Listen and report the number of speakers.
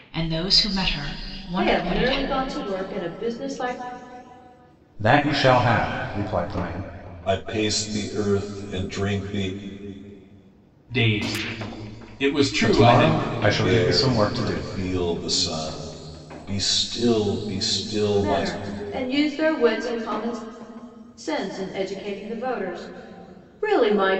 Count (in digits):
5